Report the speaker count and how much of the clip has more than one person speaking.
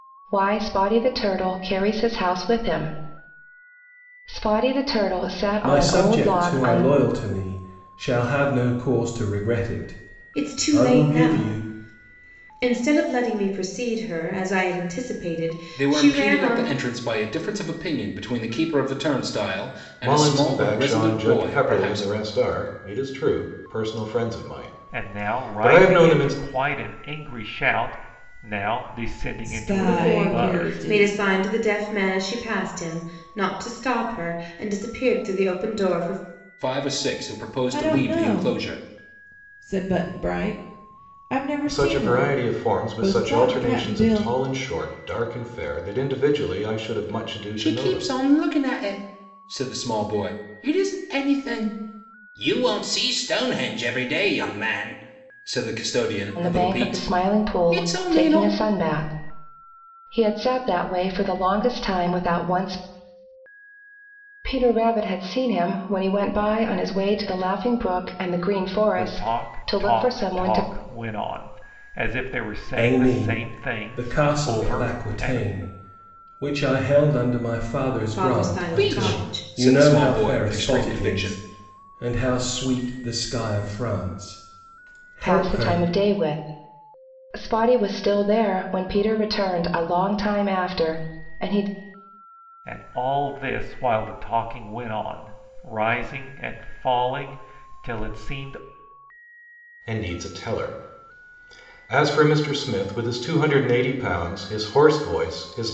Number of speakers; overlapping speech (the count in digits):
7, about 23%